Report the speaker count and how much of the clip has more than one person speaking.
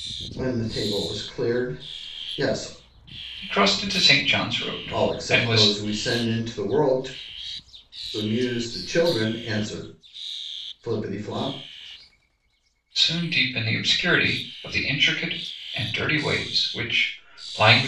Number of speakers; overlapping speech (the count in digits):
2, about 4%